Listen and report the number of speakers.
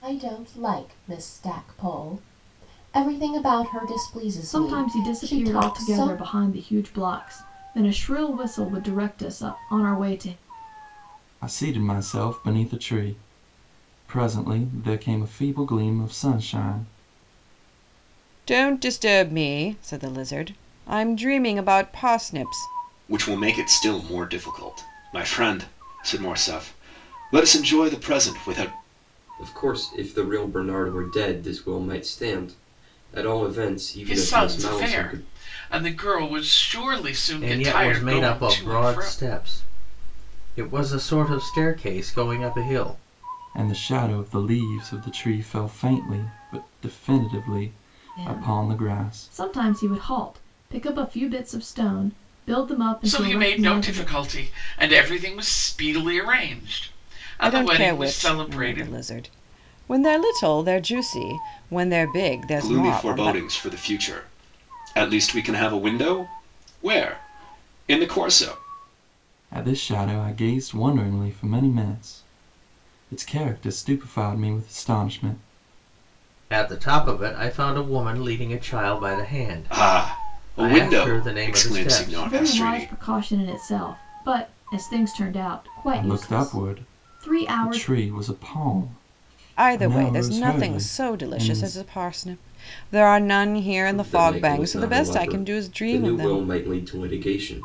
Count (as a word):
eight